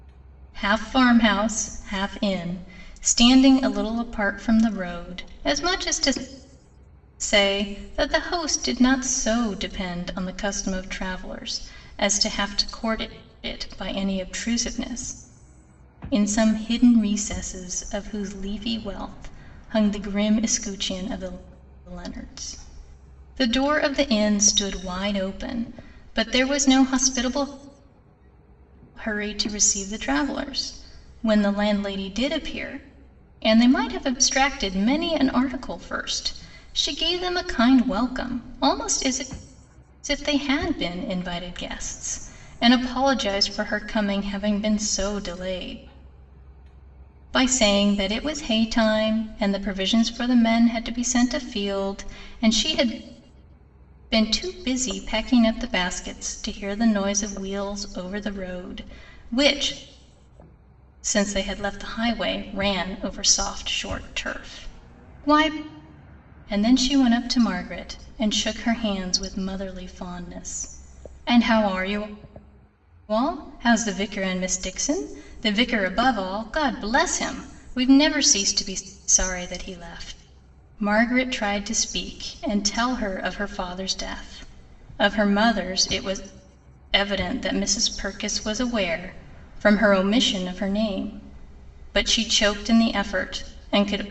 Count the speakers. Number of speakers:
1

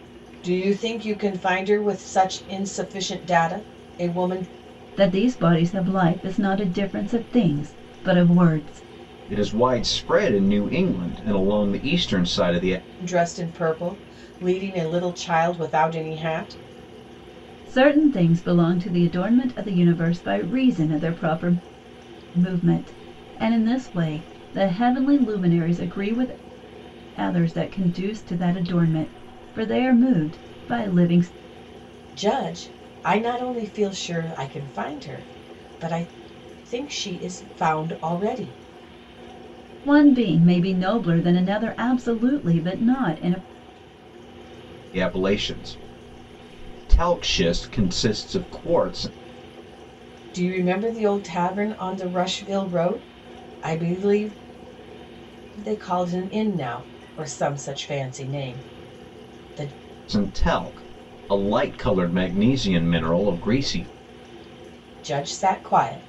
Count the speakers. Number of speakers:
3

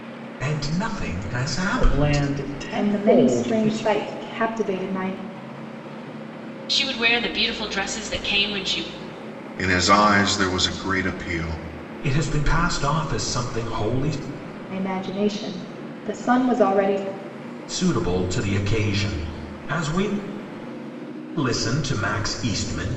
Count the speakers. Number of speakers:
5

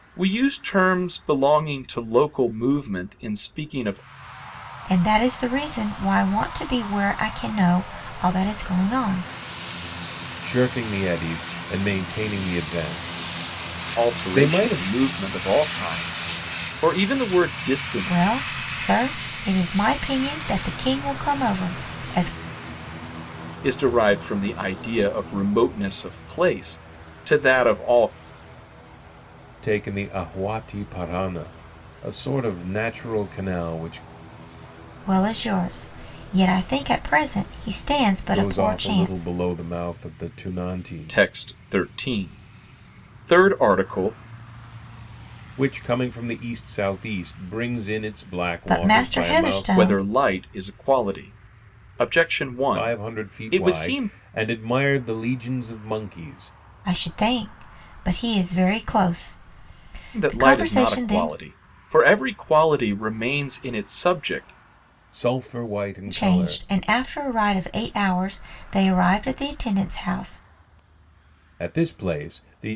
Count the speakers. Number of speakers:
3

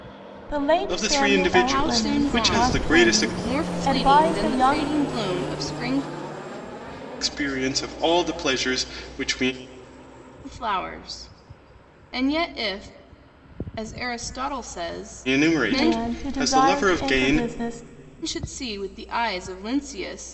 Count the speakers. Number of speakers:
3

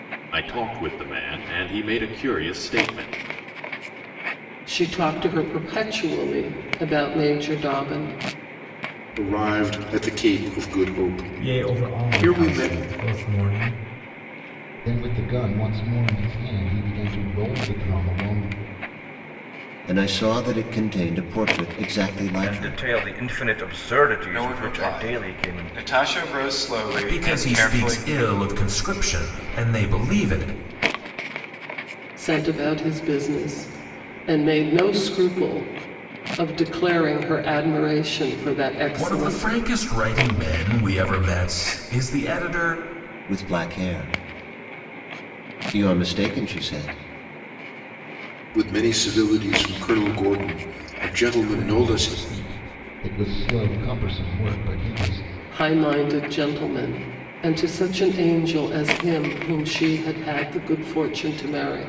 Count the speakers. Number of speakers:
9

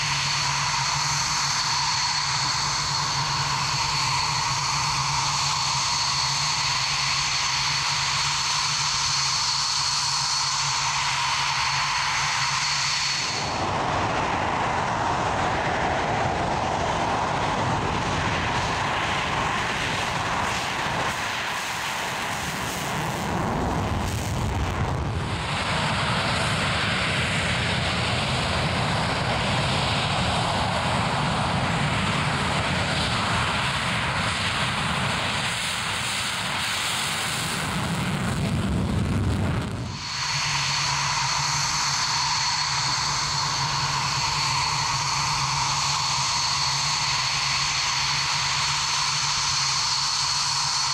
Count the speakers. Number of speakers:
0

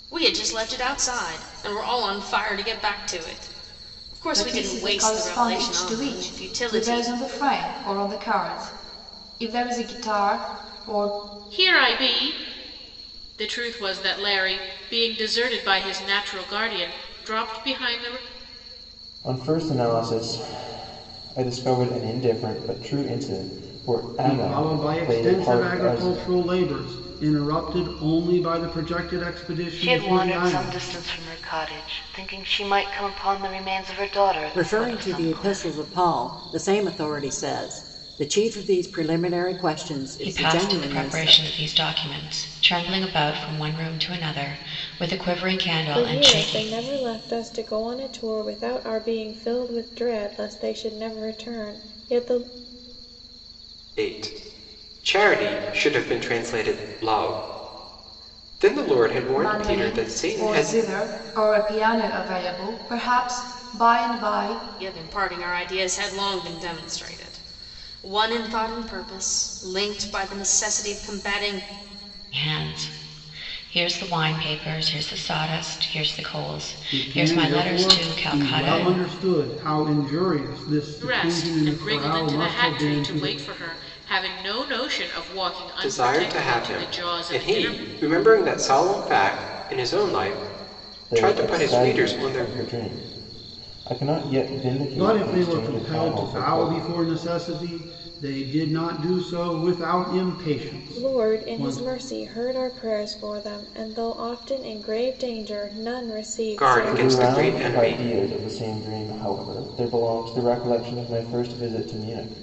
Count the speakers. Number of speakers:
10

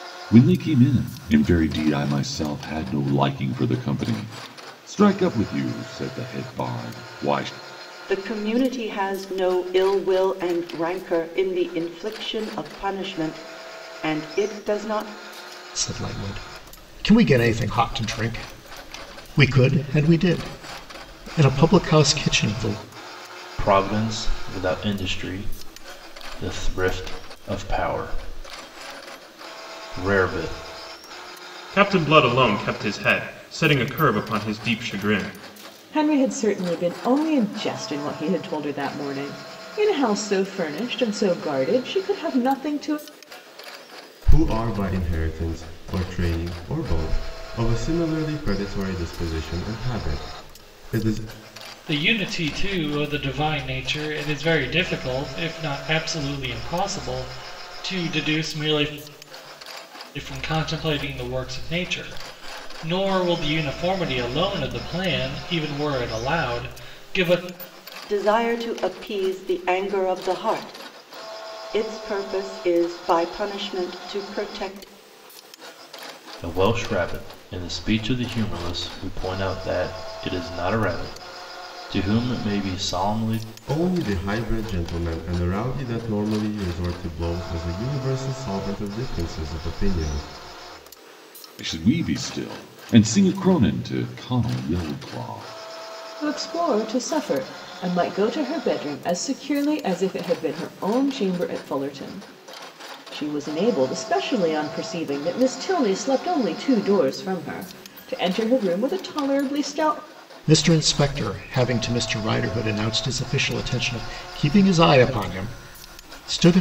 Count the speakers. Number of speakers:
8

